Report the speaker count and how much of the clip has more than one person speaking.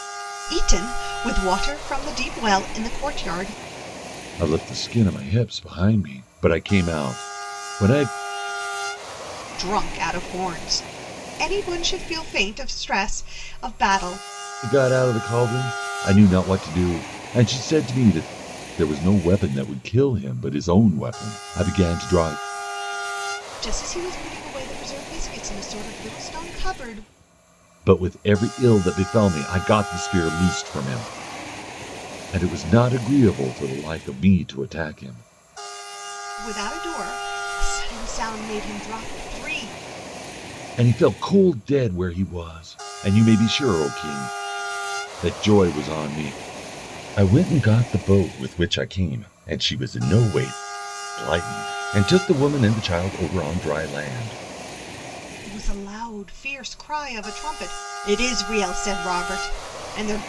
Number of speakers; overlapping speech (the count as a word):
two, no overlap